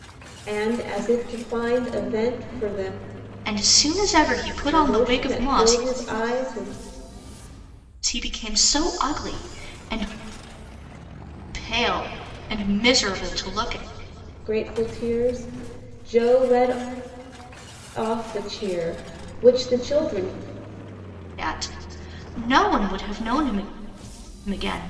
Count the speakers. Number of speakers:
2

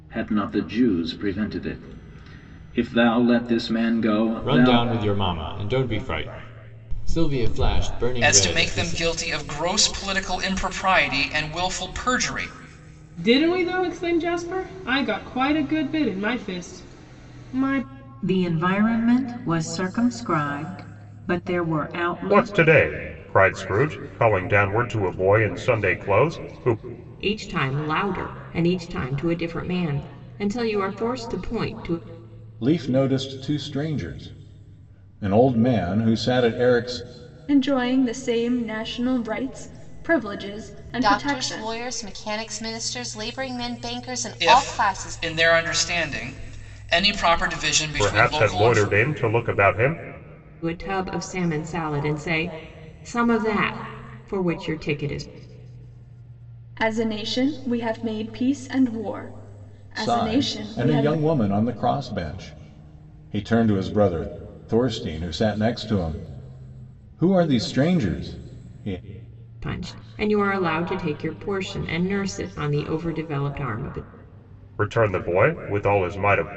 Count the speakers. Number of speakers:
10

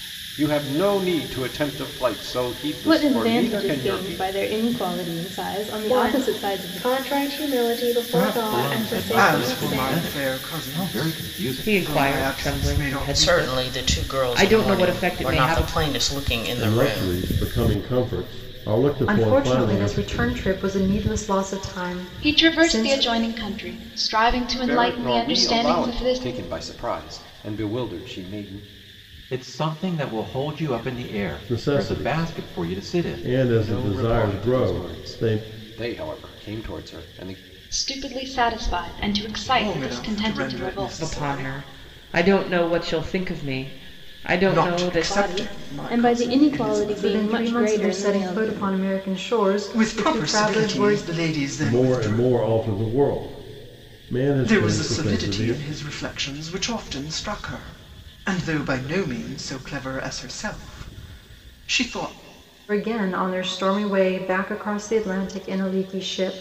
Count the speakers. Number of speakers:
10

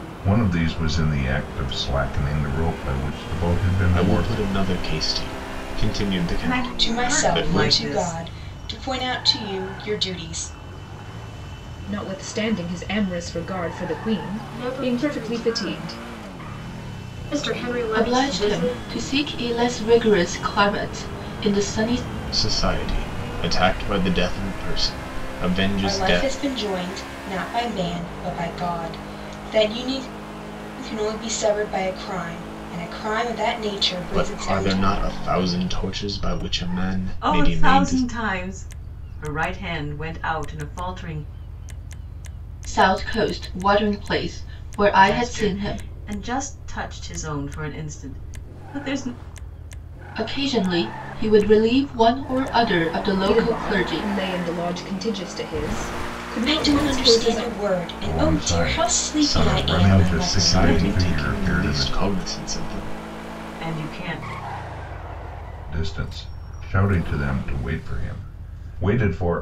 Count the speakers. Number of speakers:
7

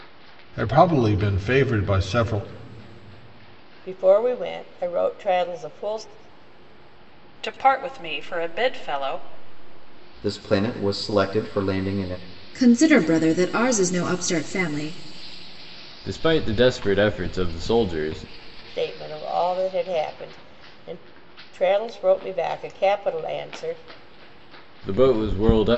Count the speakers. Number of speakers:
6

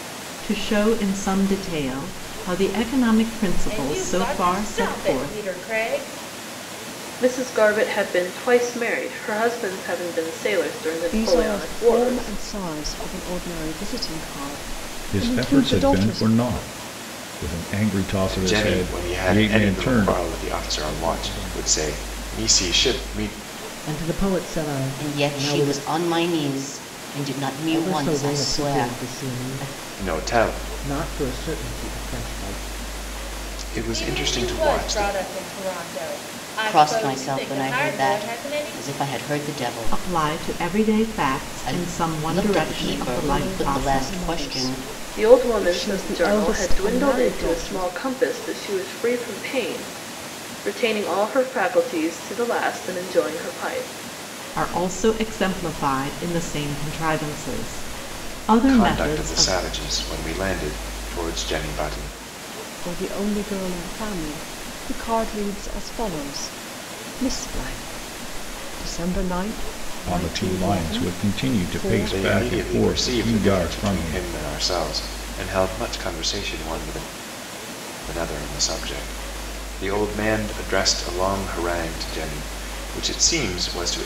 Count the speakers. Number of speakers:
8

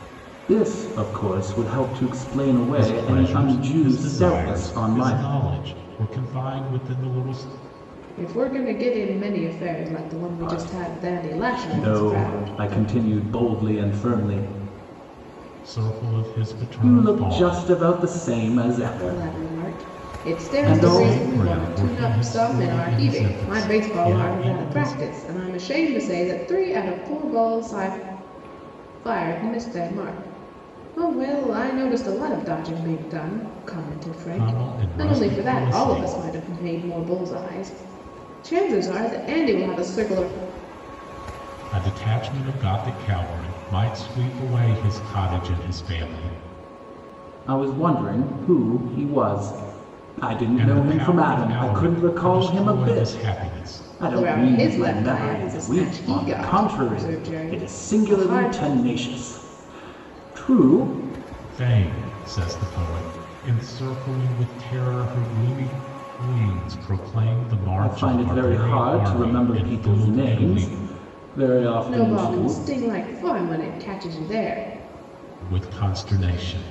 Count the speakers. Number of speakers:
3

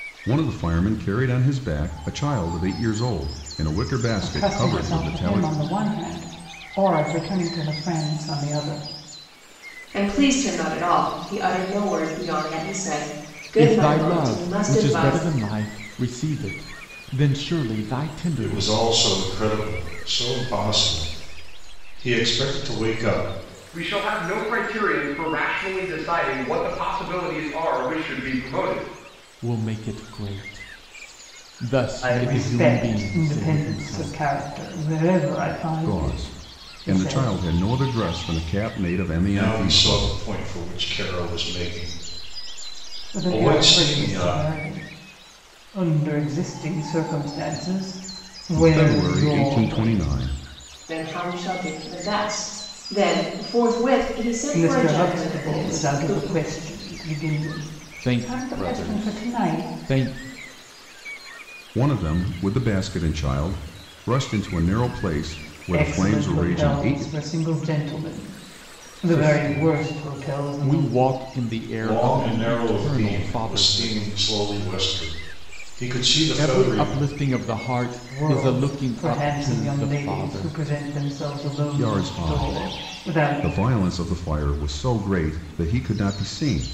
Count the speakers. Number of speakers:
6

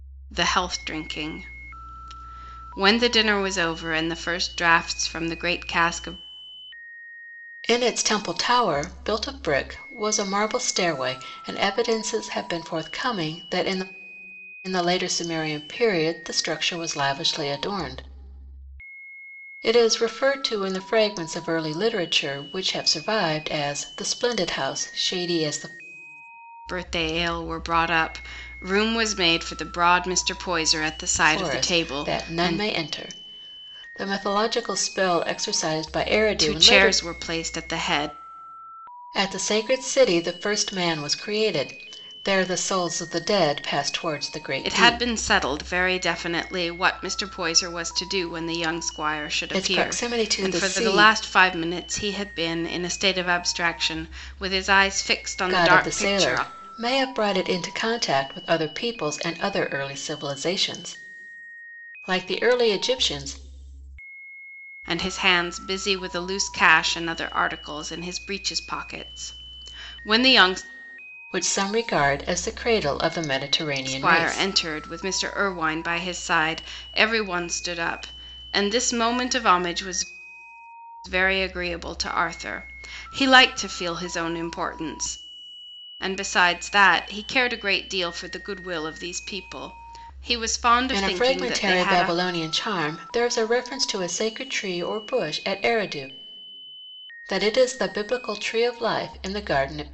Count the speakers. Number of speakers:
2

